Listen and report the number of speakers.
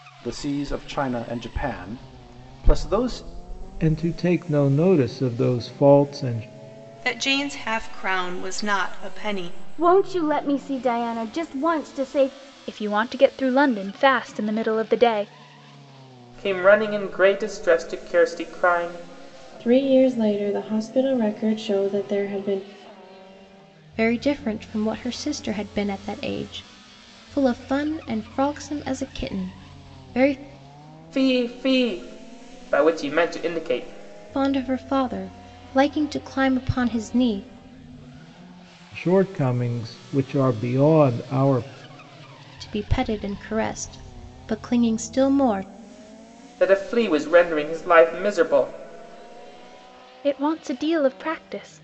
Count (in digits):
8